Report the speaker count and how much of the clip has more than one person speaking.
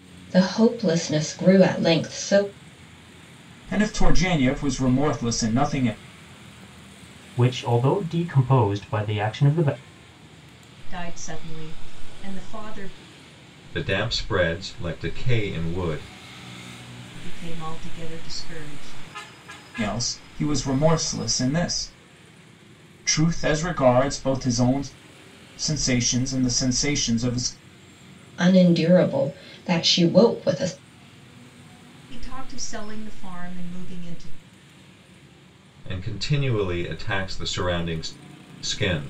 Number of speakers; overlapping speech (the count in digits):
5, no overlap